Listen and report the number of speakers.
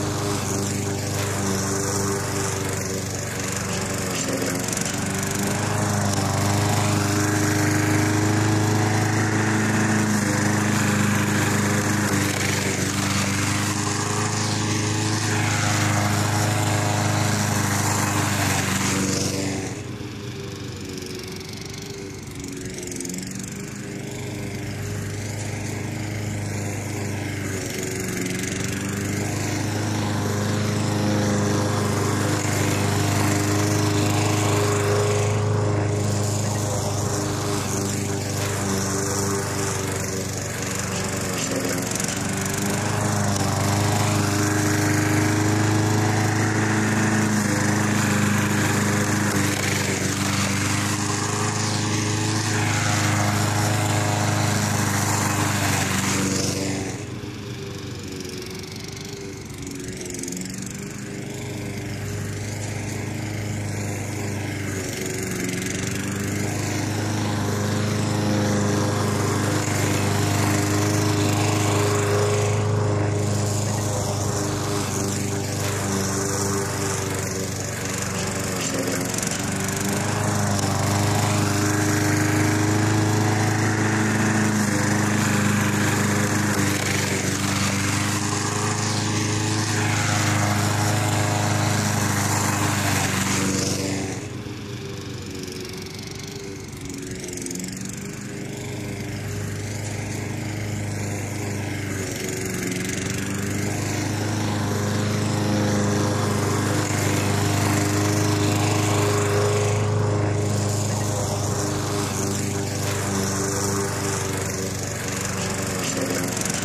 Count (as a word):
zero